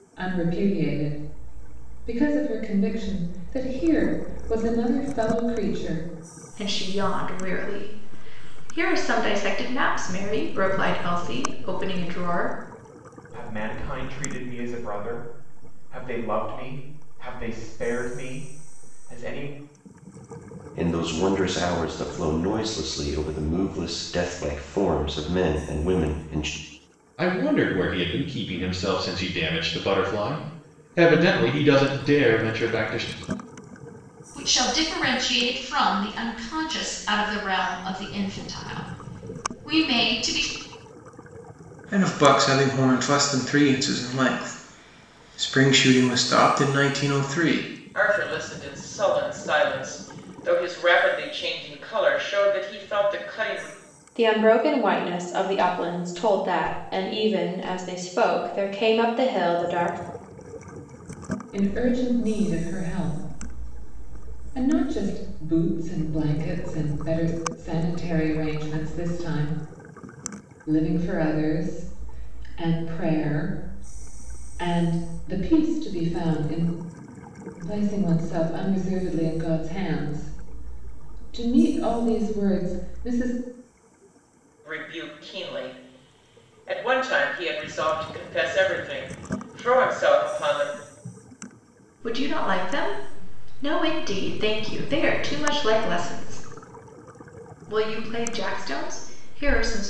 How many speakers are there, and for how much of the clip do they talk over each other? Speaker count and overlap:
9, no overlap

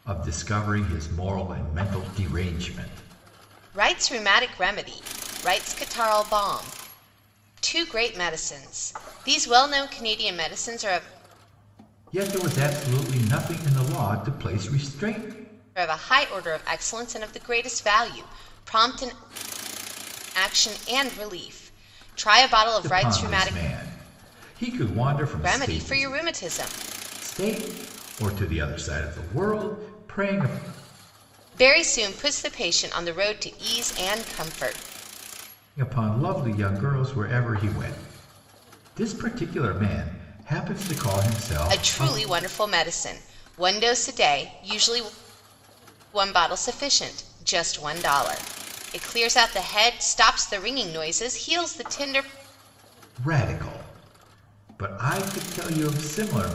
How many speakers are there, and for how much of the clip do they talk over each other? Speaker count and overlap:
2, about 3%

